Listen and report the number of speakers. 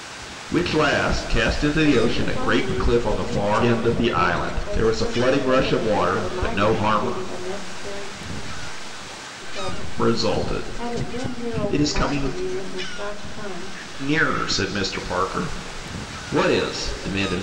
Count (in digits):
2